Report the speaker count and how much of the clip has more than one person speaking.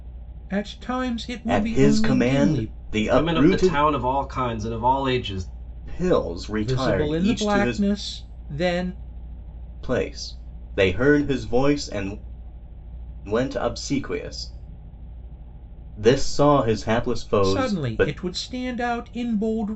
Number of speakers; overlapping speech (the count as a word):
three, about 21%